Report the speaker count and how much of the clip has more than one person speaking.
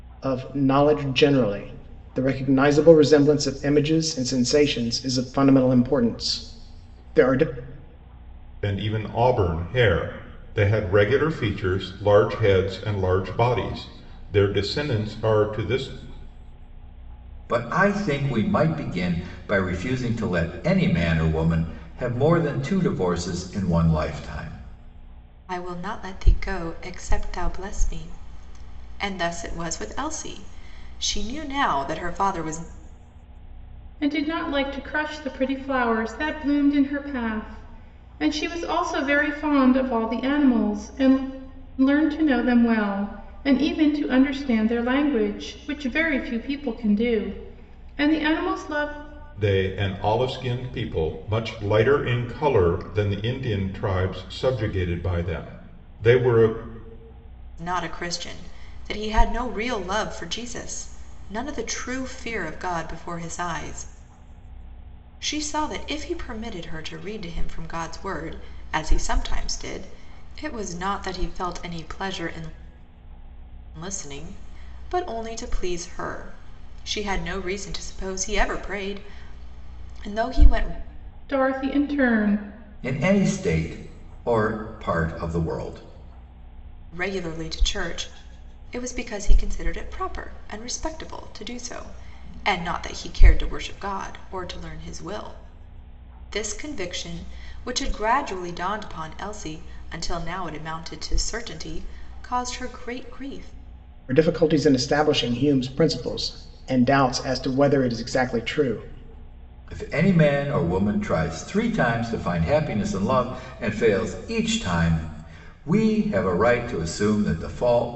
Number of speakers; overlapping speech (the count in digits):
5, no overlap